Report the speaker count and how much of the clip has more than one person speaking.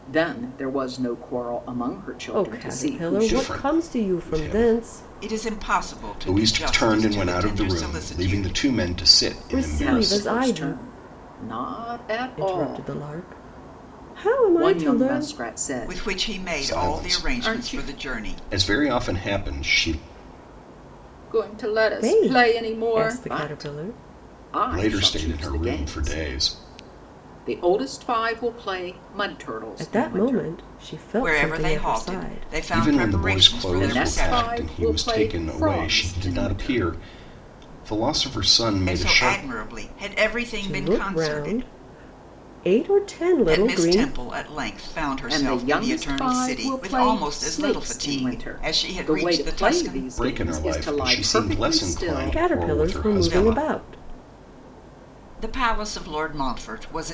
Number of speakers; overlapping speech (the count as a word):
four, about 56%